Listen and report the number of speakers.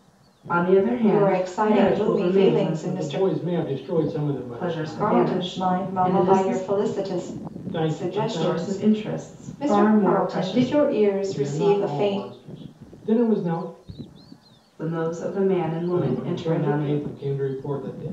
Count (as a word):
three